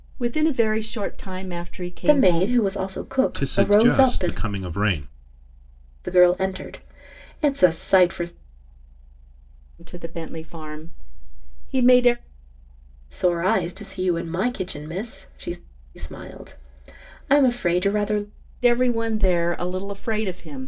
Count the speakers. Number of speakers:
3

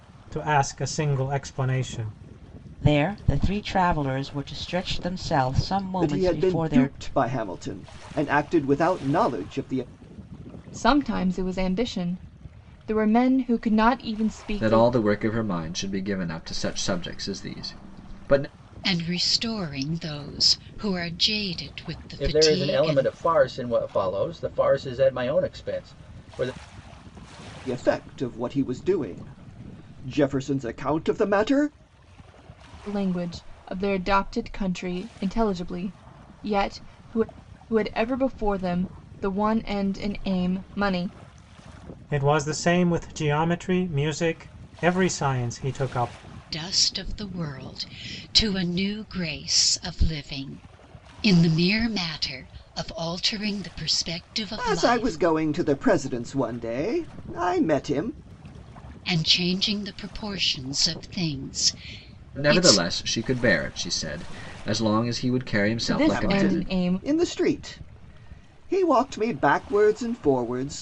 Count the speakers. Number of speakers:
7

